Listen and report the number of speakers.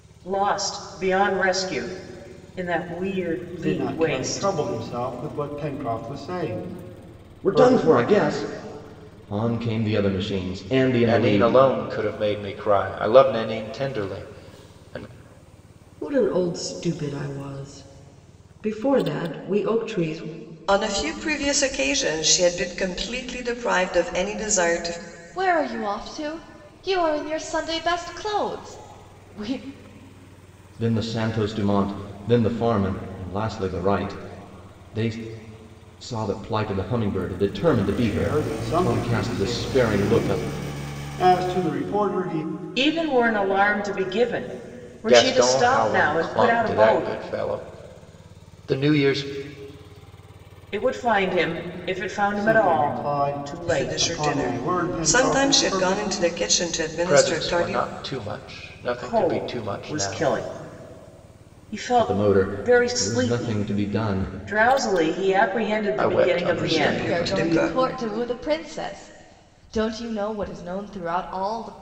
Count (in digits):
7